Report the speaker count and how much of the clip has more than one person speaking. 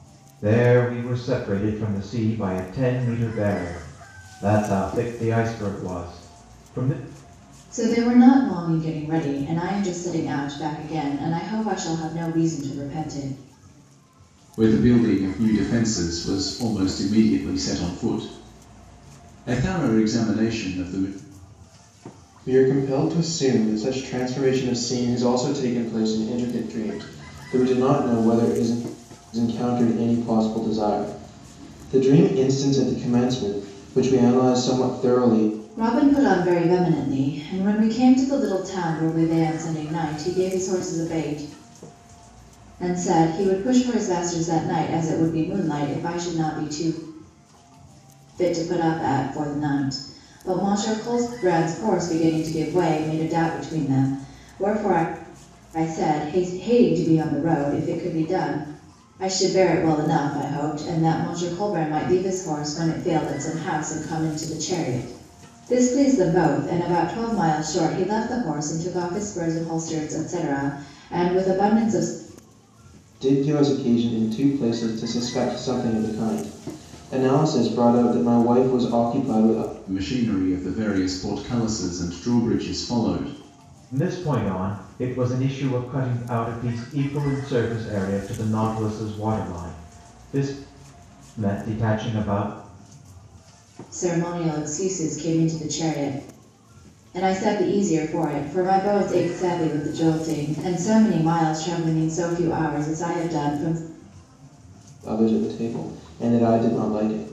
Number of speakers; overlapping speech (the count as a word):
four, no overlap